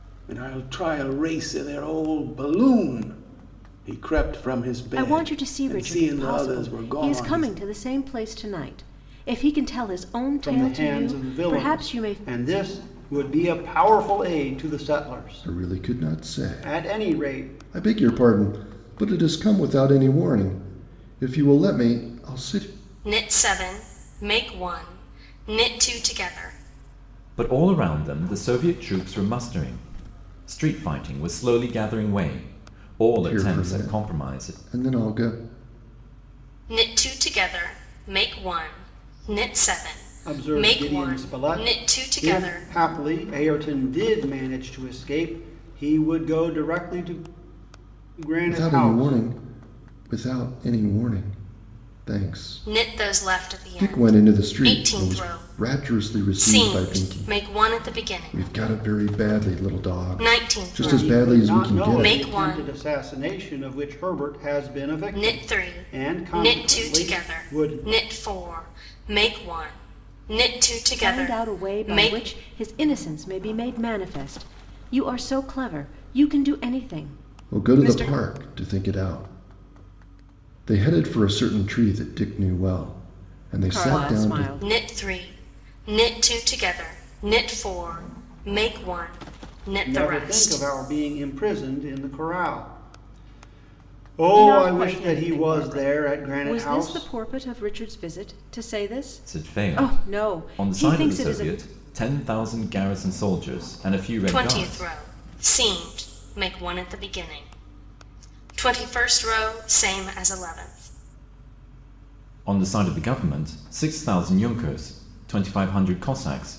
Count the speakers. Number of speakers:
six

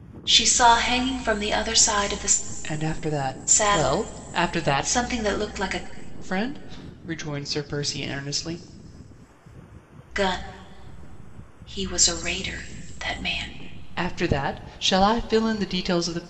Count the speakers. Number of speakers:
two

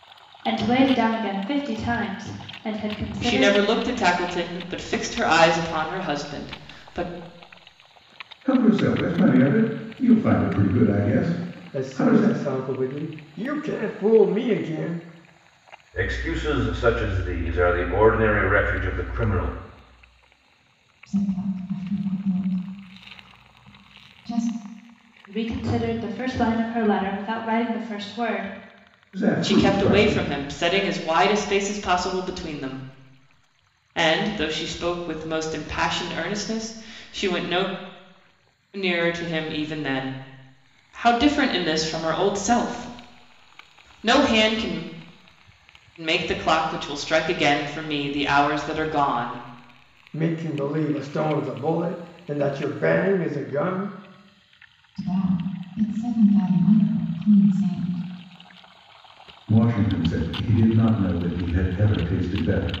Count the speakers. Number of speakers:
six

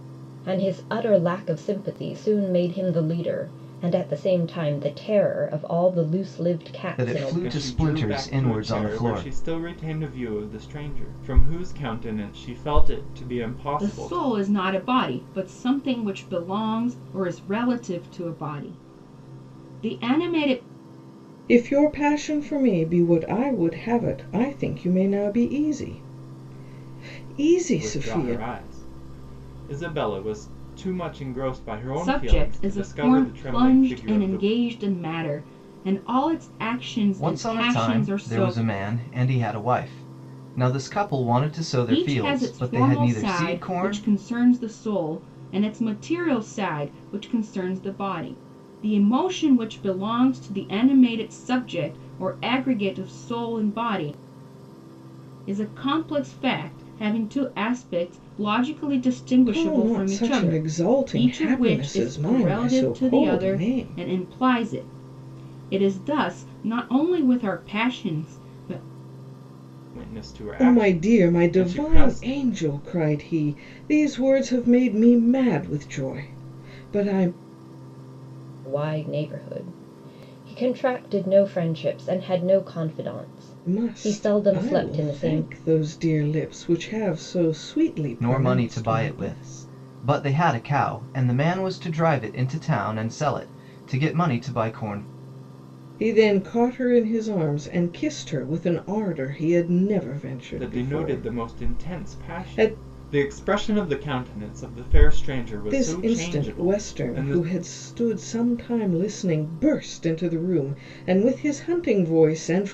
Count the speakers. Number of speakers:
five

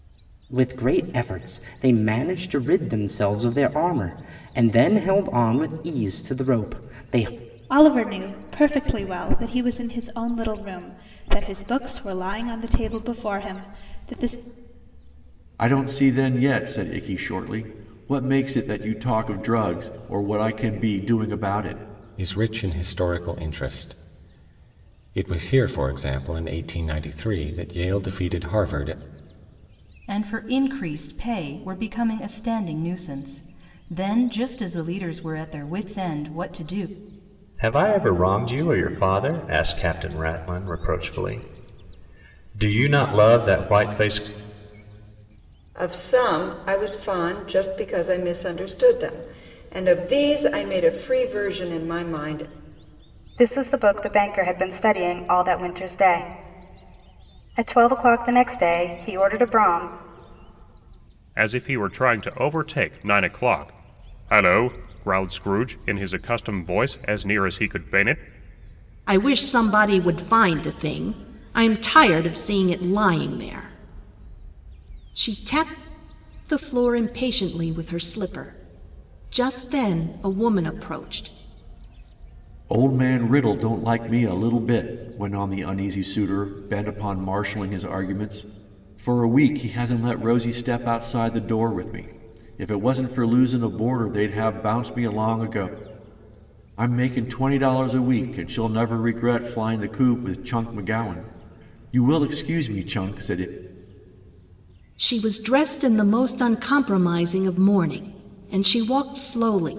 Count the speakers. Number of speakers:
ten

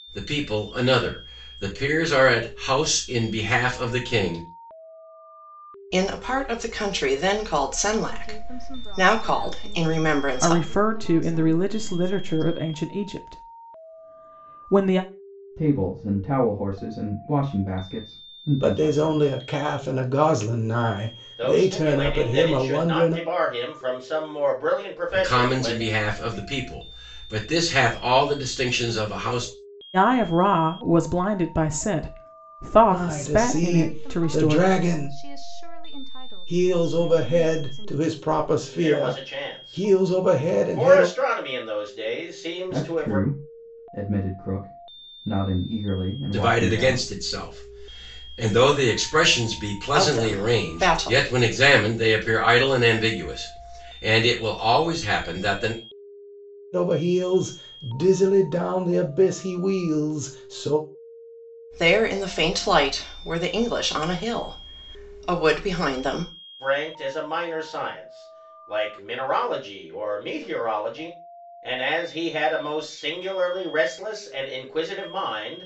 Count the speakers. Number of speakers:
seven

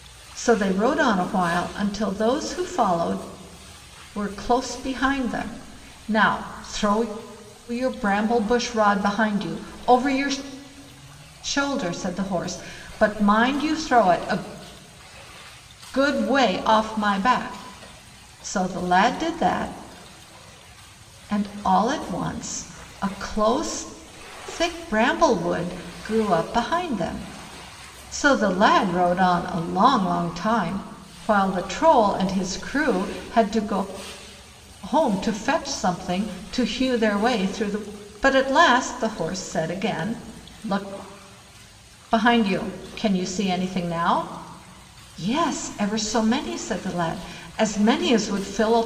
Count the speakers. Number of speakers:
one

